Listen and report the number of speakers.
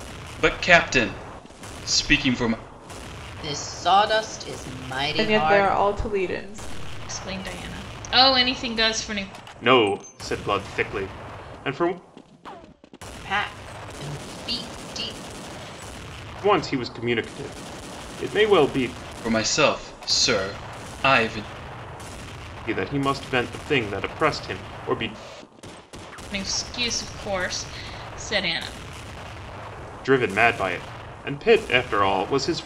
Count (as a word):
five